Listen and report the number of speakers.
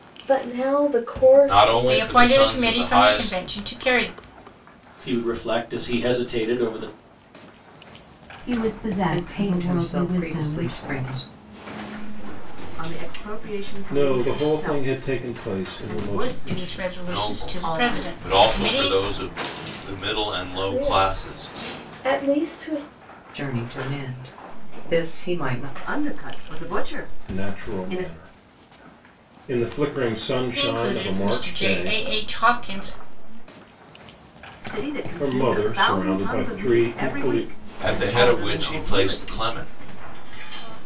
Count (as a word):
nine